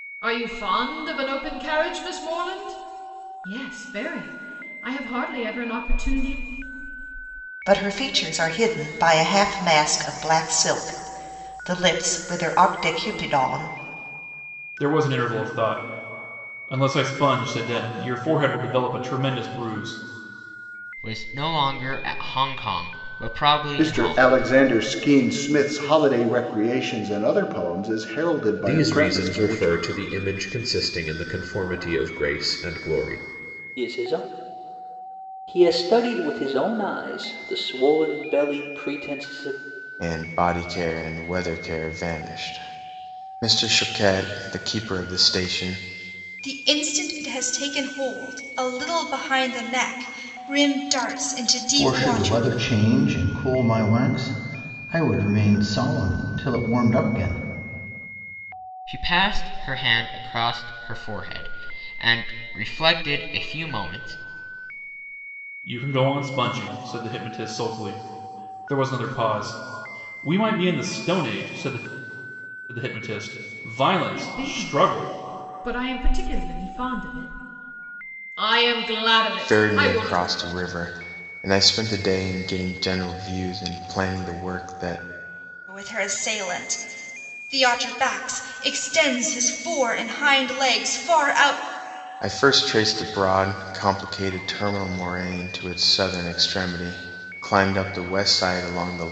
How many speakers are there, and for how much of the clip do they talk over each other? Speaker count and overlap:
10, about 5%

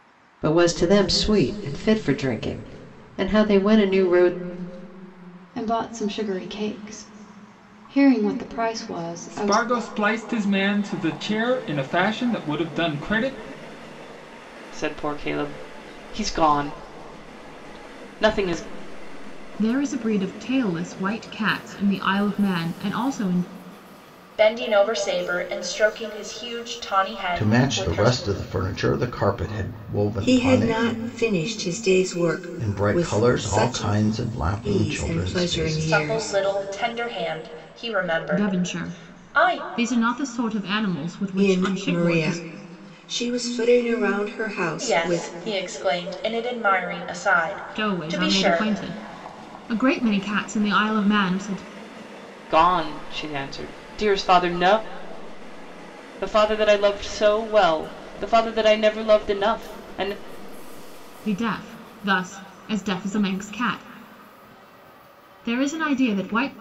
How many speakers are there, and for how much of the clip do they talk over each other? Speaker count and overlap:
8, about 13%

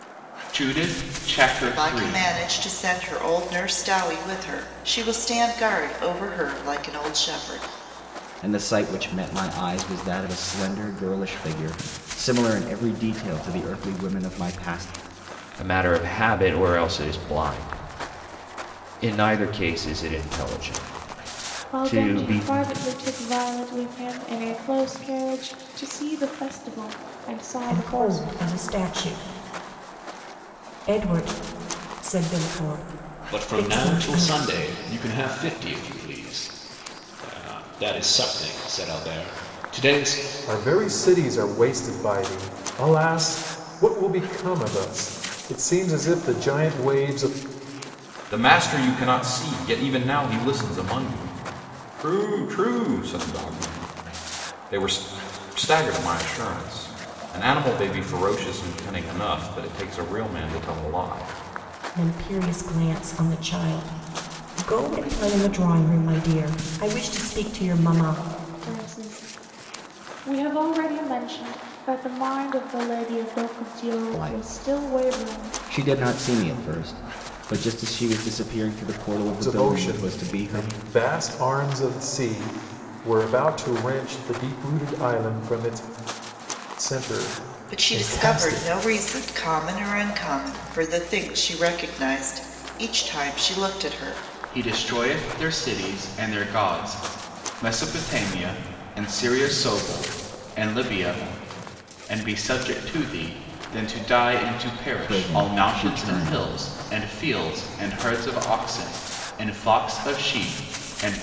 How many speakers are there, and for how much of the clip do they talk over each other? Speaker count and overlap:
9, about 8%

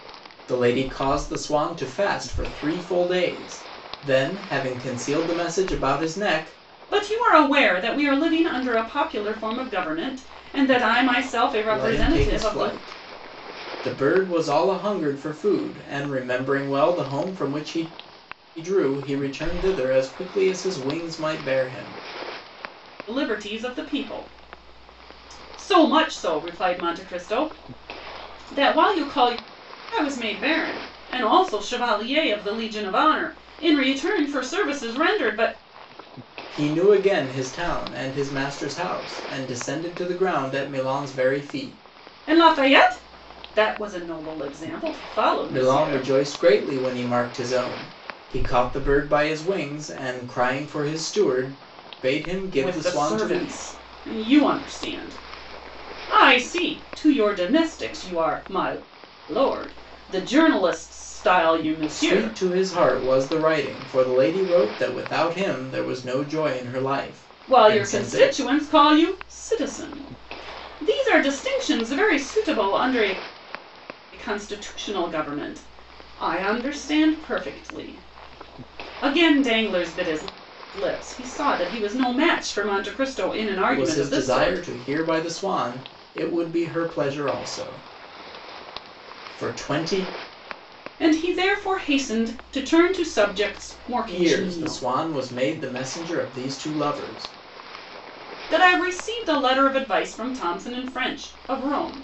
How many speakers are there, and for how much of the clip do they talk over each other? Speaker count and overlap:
2, about 6%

